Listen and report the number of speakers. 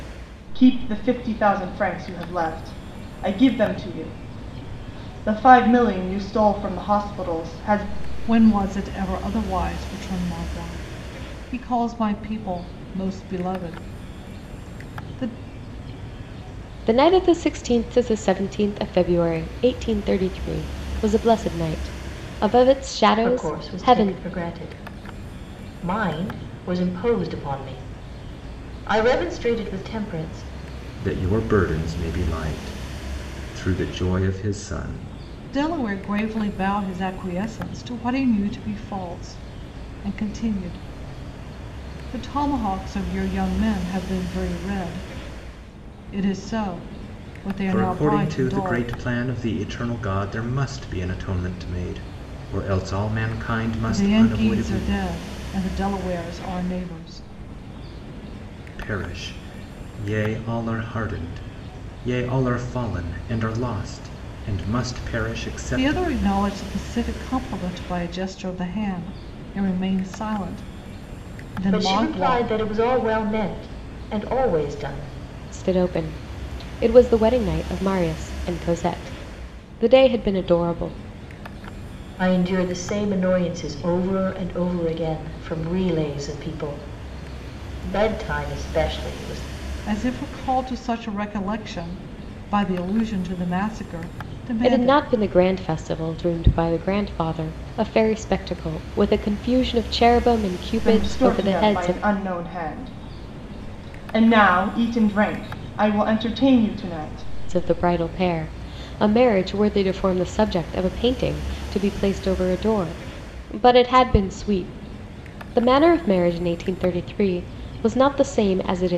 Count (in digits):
5